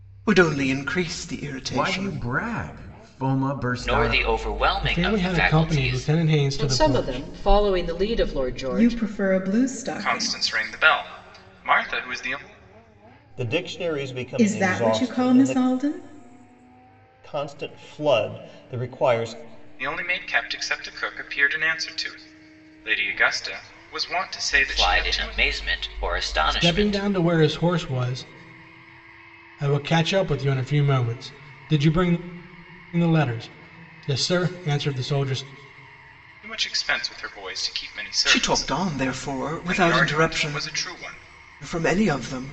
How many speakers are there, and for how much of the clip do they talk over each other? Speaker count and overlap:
8, about 19%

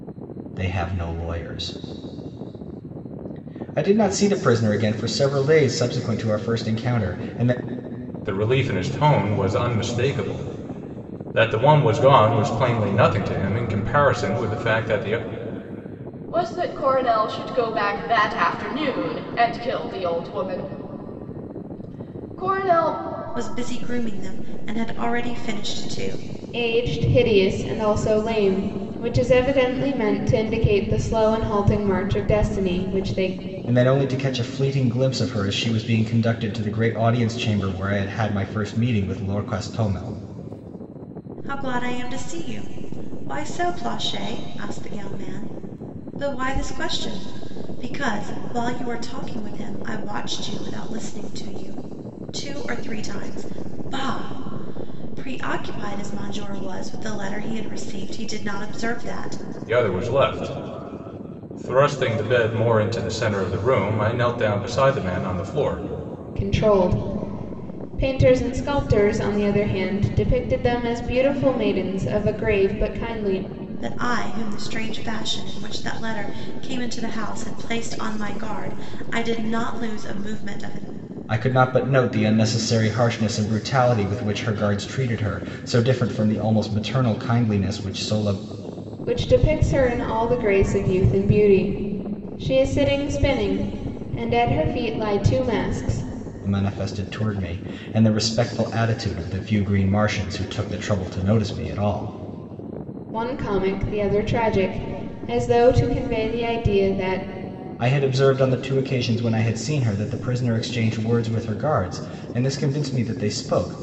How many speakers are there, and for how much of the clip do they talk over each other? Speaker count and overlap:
5, no overlap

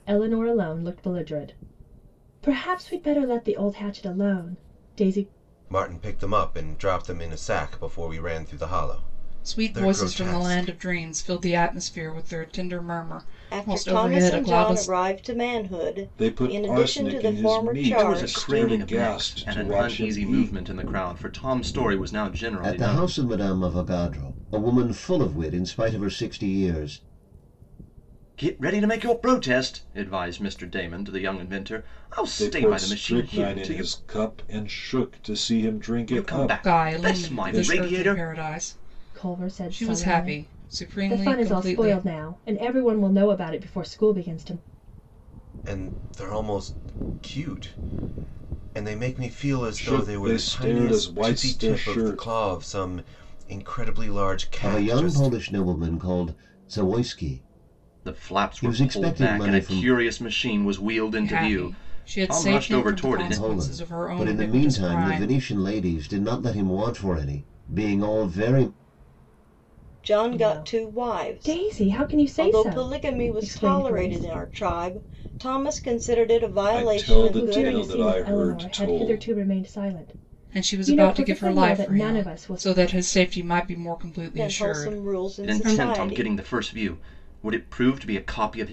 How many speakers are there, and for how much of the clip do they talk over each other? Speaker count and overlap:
7, about 38%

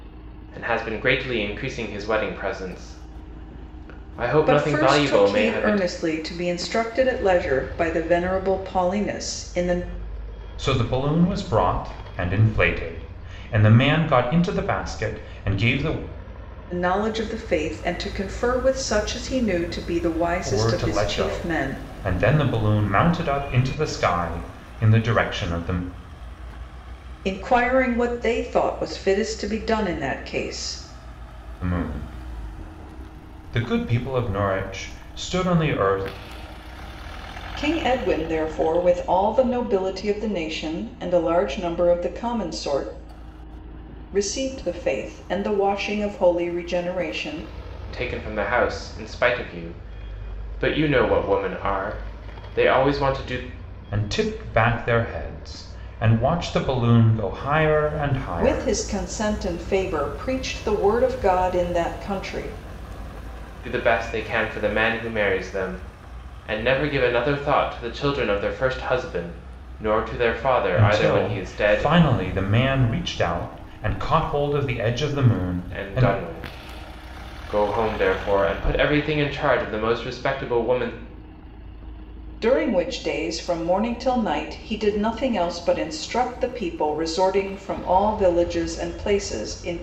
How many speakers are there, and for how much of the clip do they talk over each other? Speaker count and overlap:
3, about 5%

